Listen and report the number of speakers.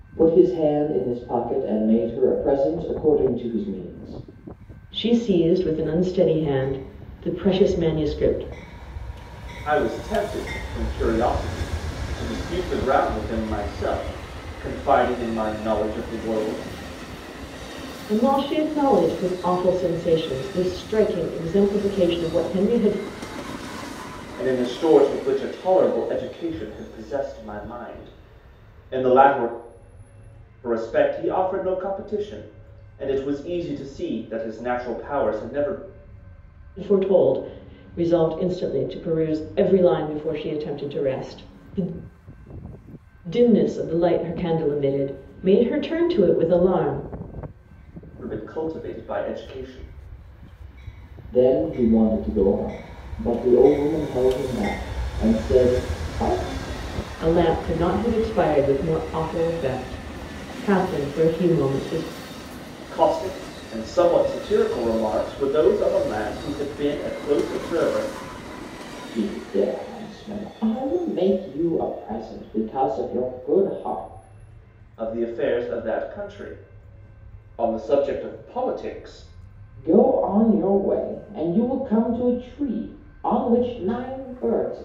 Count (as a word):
three